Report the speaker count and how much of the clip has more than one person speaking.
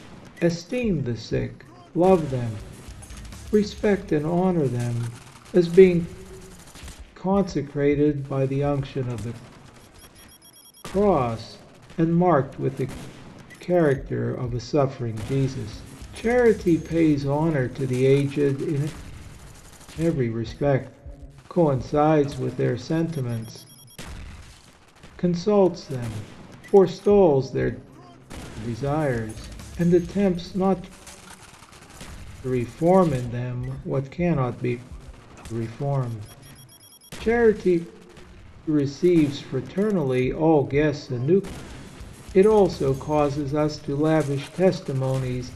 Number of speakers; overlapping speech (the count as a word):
one, no overlap